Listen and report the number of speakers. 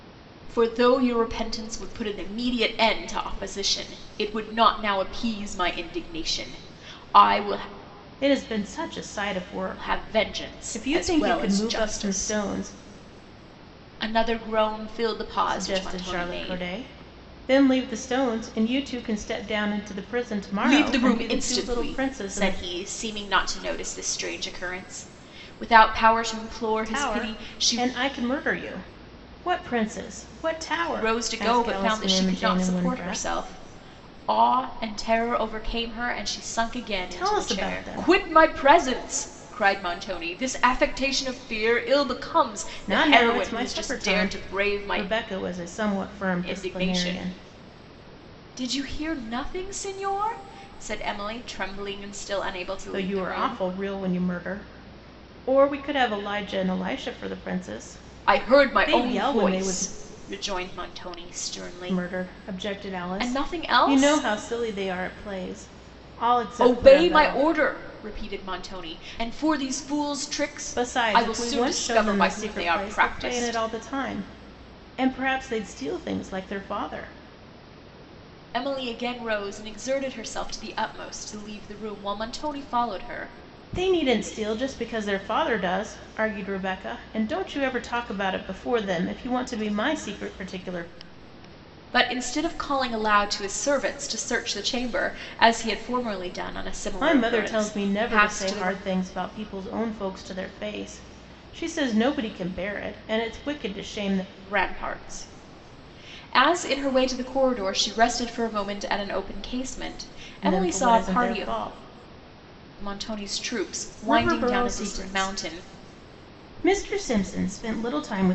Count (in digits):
2